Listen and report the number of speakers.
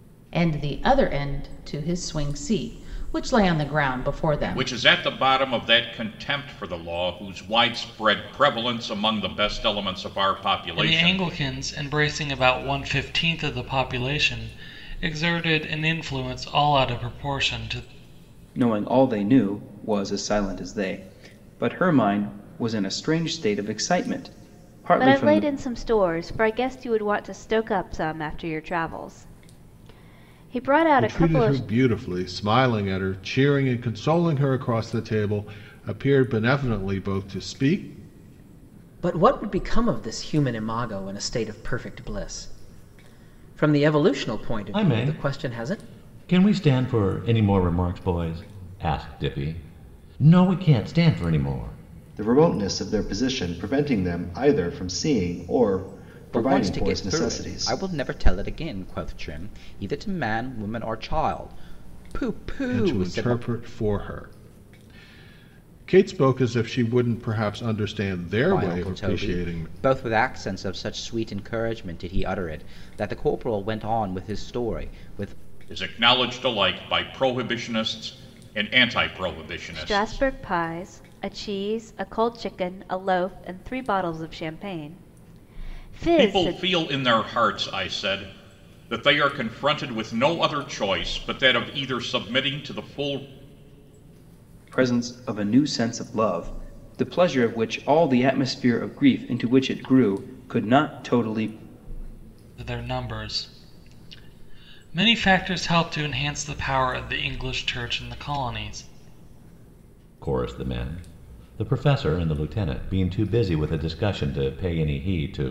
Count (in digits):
10